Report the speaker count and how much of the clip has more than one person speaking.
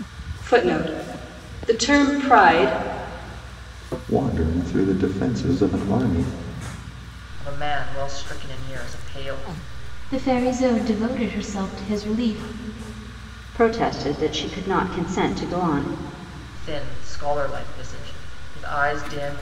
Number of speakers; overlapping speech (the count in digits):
5, no overlap